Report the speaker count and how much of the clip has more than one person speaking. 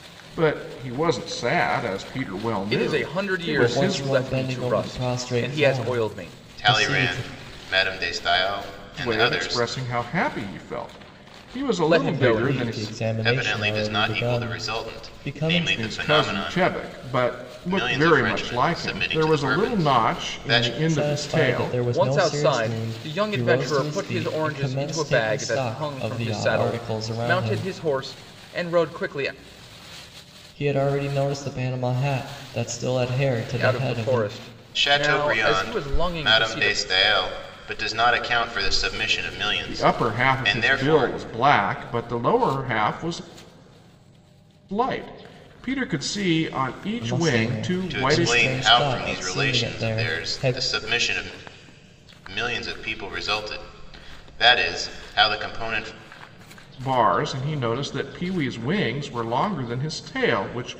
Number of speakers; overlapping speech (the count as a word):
four, about 45%